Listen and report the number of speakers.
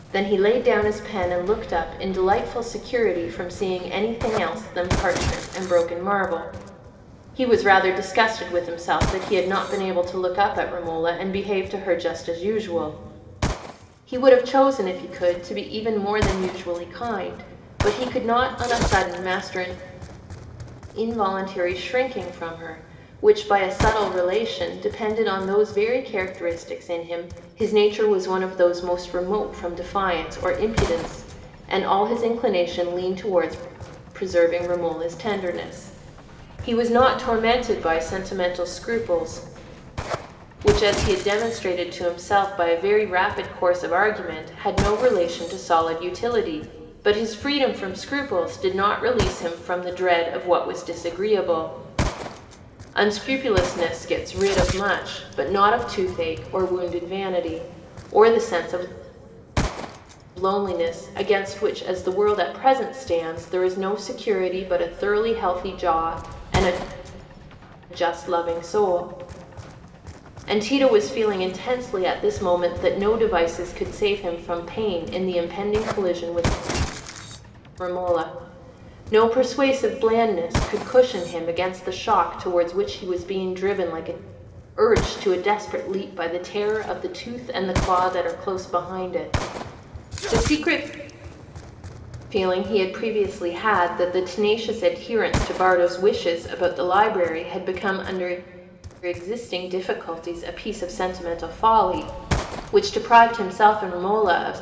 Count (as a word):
one